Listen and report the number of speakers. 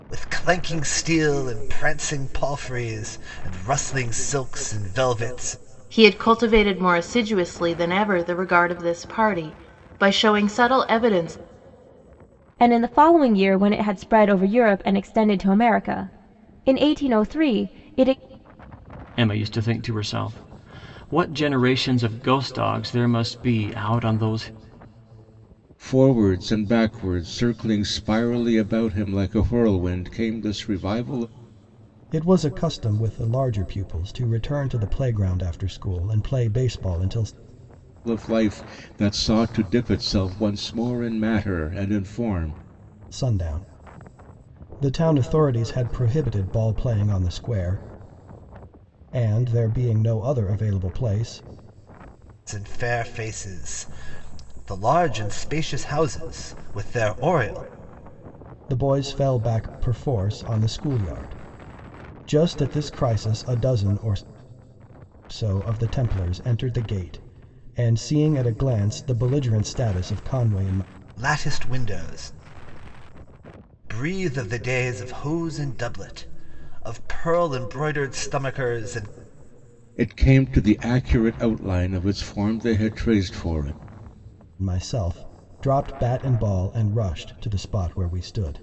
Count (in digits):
6